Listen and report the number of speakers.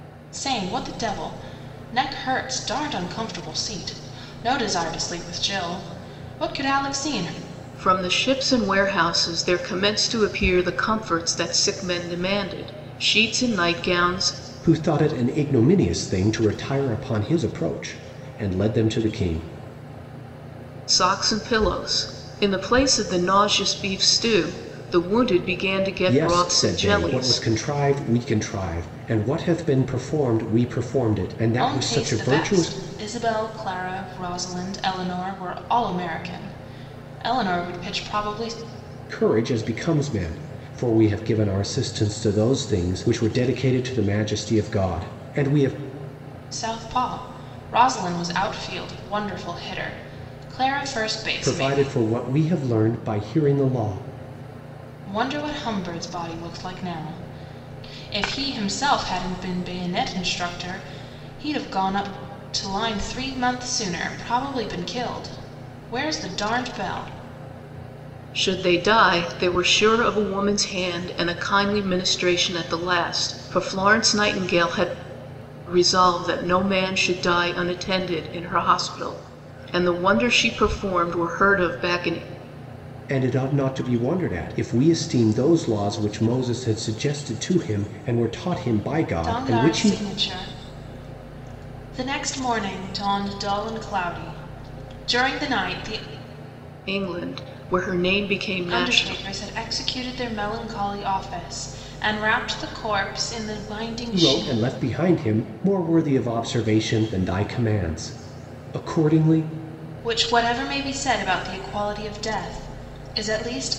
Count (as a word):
three